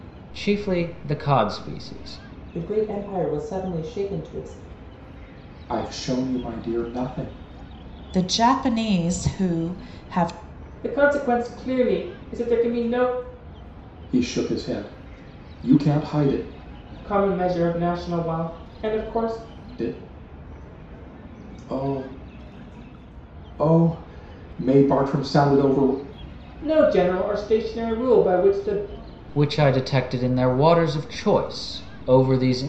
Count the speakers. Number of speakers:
five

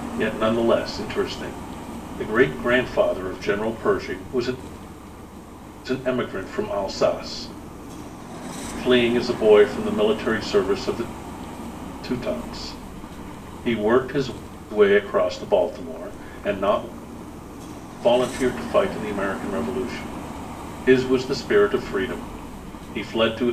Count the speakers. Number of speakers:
one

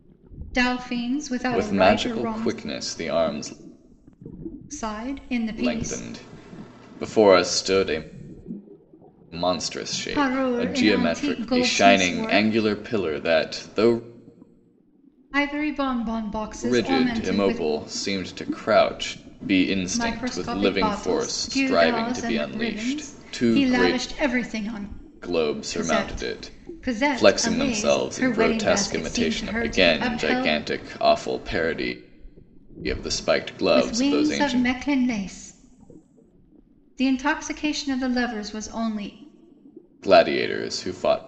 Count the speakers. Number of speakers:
two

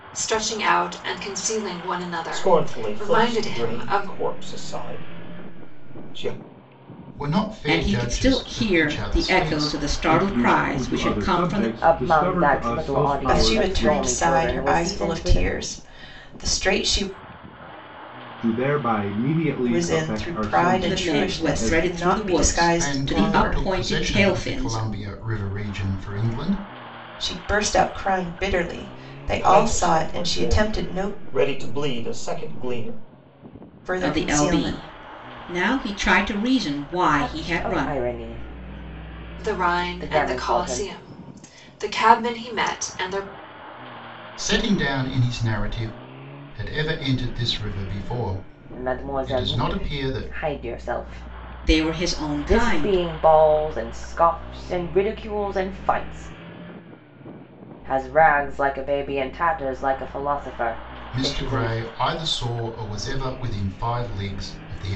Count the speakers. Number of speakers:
seven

